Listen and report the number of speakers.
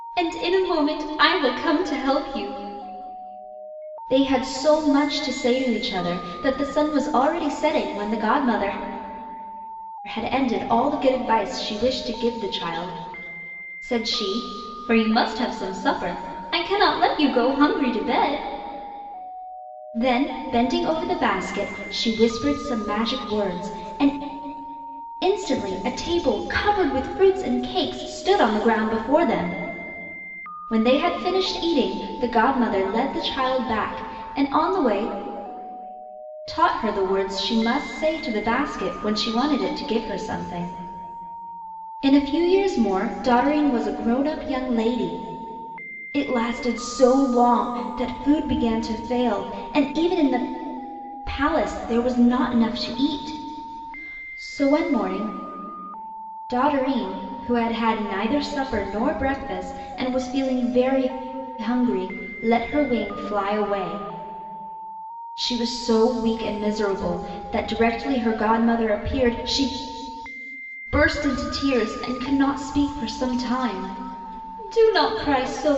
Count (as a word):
one